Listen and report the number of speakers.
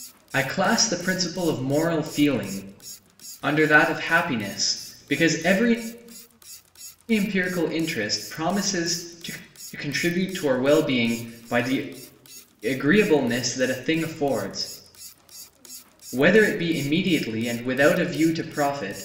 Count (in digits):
1